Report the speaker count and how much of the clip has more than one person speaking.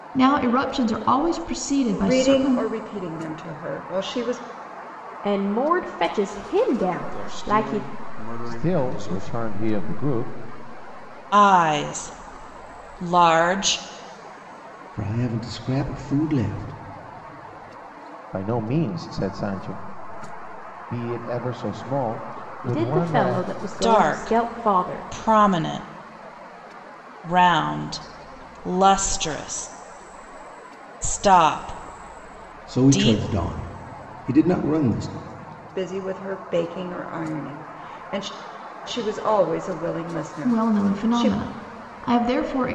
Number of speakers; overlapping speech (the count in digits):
7, about 15%